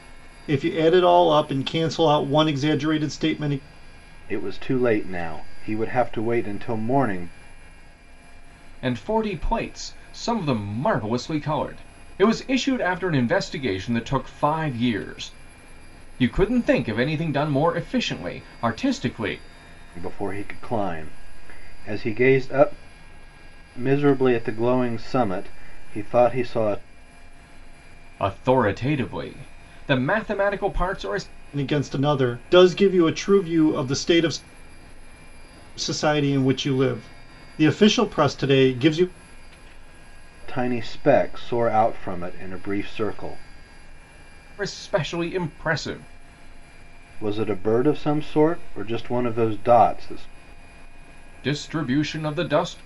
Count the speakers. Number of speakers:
3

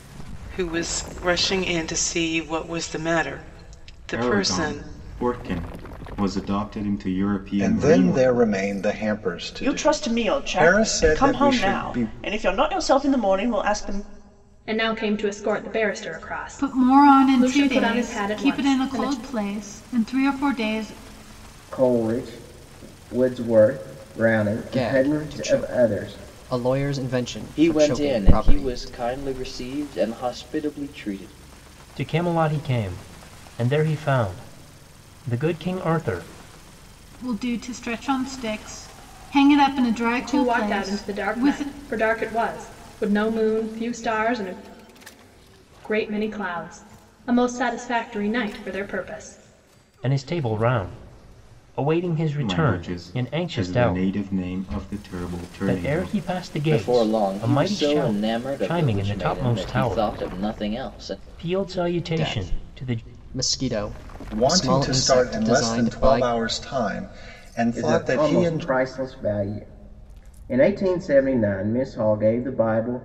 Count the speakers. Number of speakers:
10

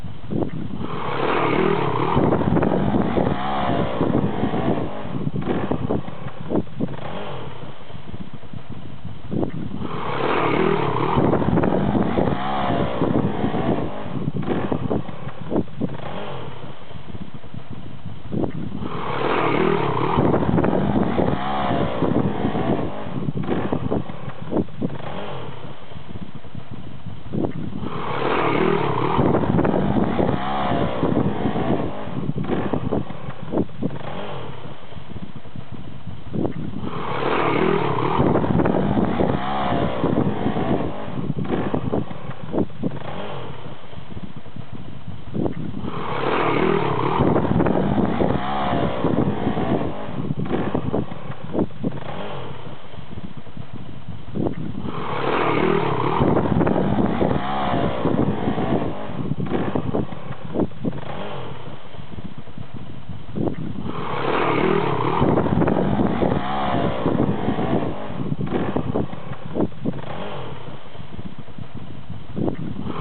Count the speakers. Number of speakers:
0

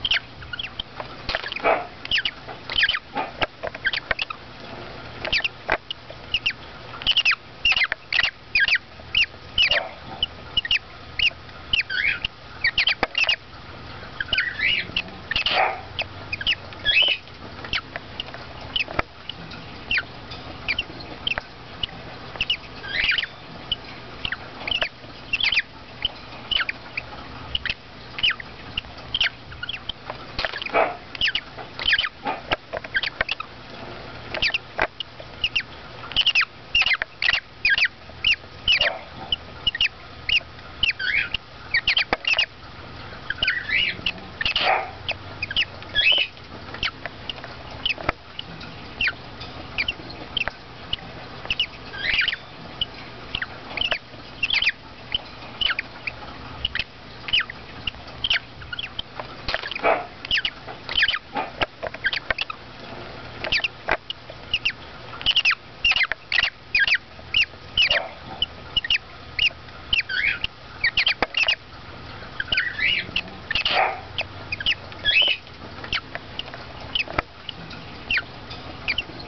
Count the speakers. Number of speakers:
0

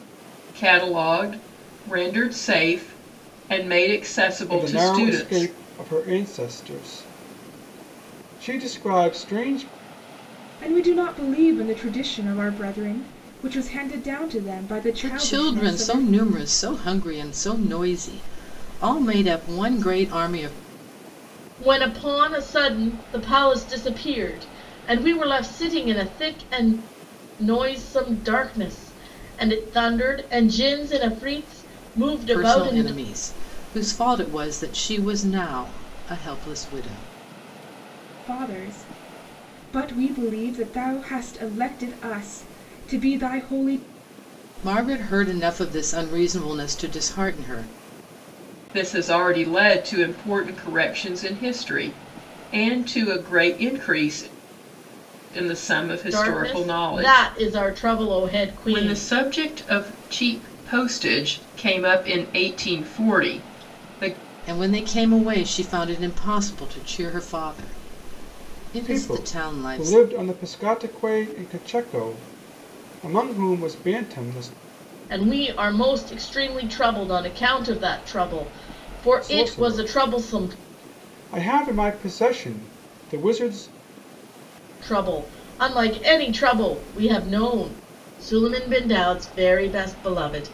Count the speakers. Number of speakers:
5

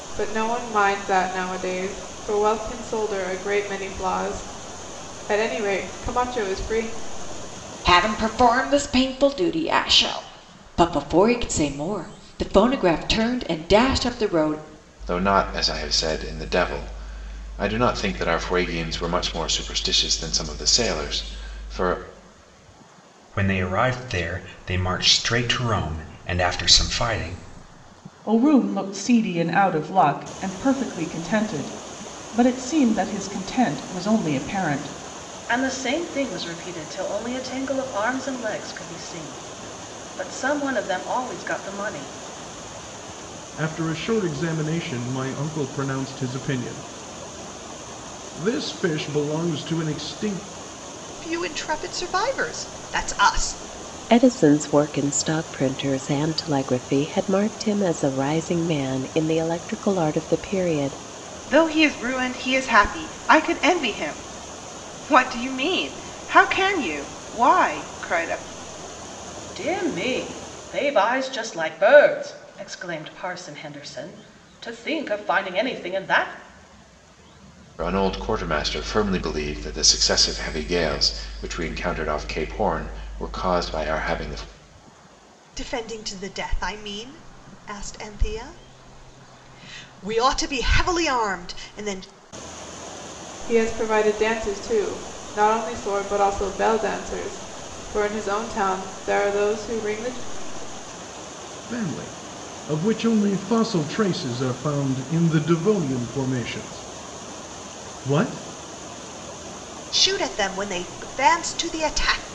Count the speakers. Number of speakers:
10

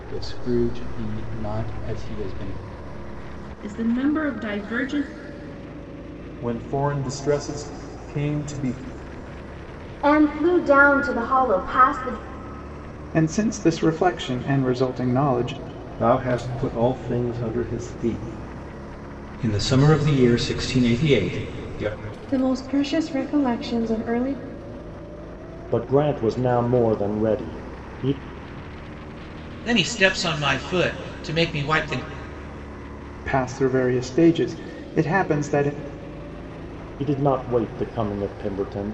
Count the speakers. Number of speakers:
10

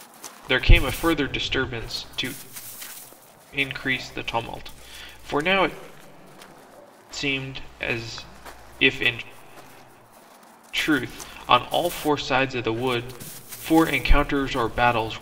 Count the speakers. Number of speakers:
1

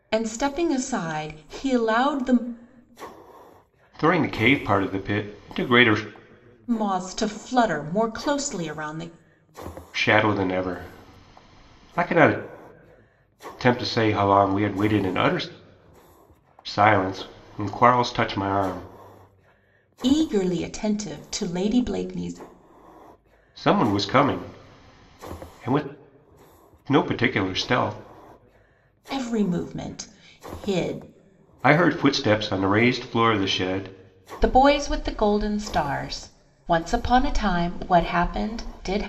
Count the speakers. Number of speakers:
2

